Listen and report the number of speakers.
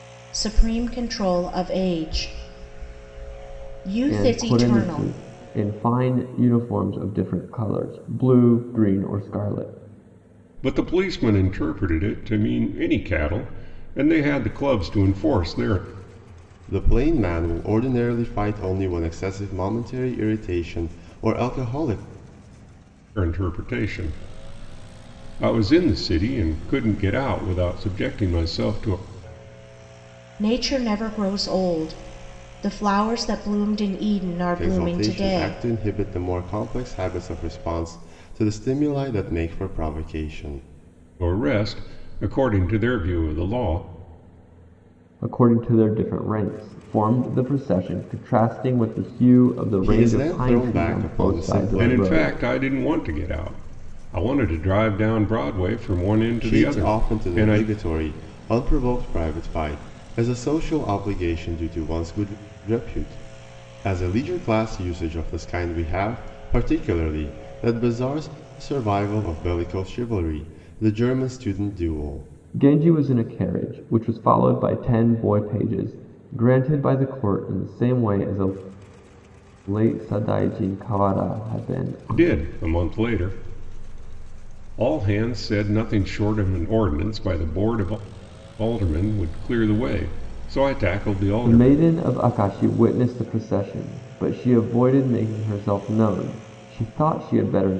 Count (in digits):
4